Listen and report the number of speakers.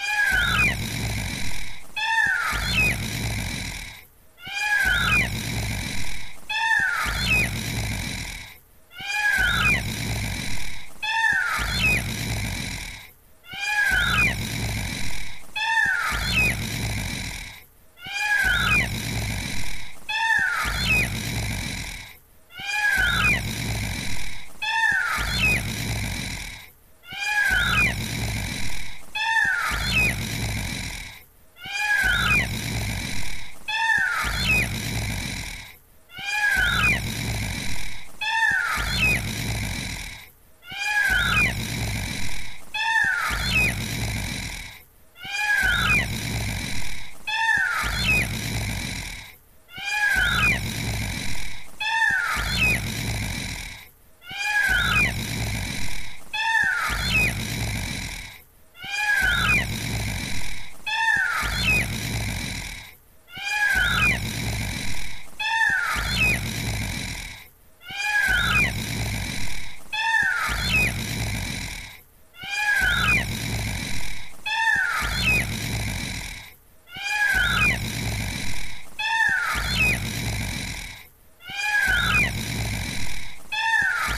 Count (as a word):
zero